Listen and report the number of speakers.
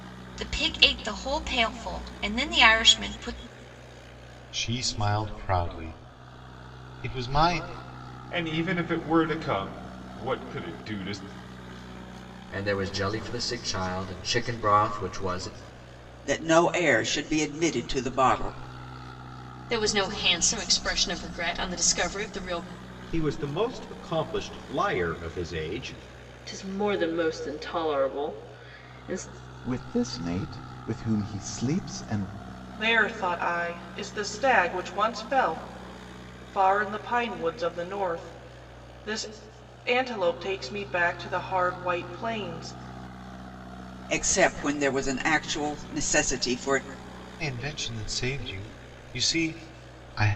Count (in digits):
10